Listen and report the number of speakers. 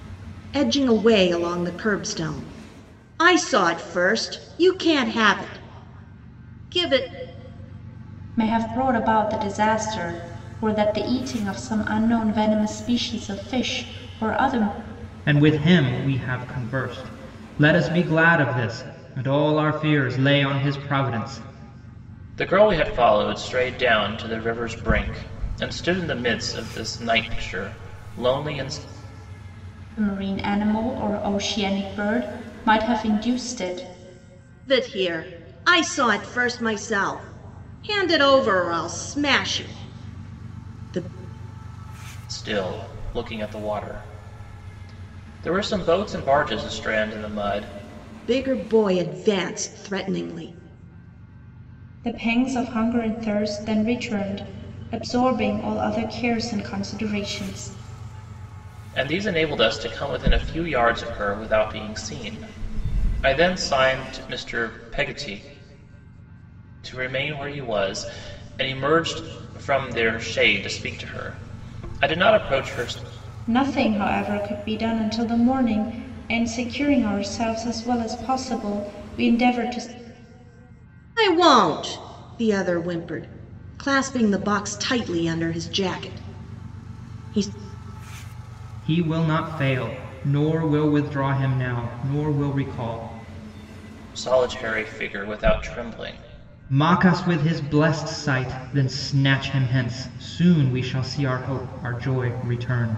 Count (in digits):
4